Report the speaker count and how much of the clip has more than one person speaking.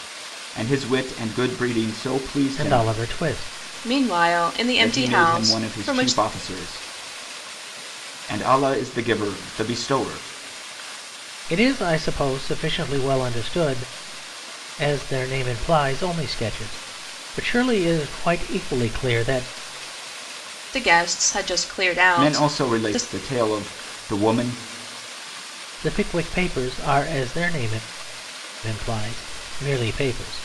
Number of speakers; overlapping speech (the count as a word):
three, about 9%